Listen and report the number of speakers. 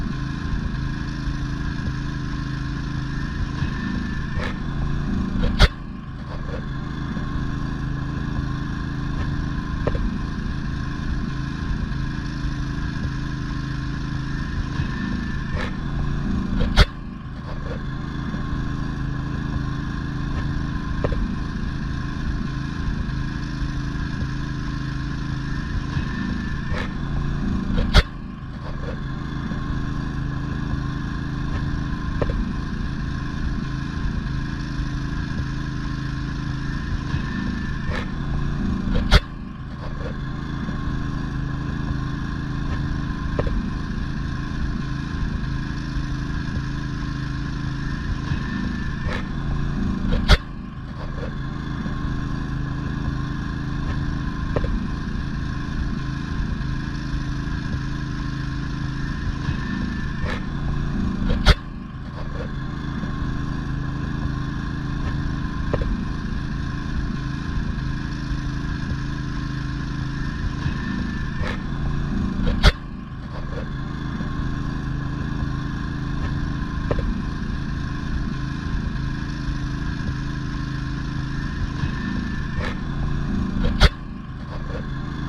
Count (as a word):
zero